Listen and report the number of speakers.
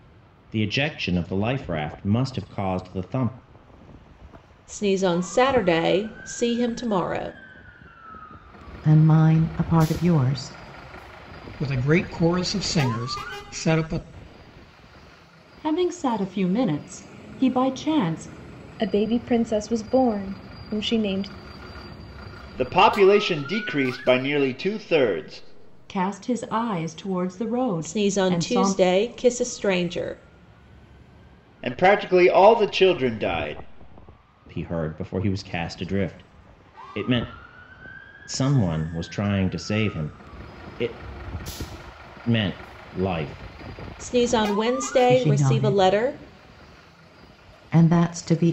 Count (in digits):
7